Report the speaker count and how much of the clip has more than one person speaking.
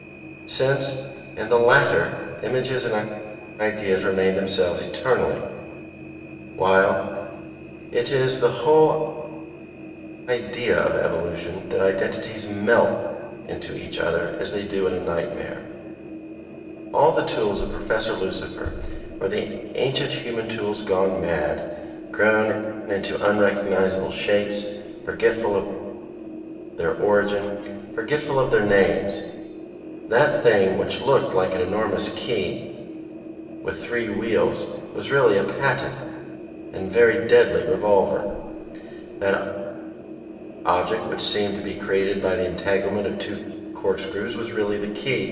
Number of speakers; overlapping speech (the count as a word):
one, no overlap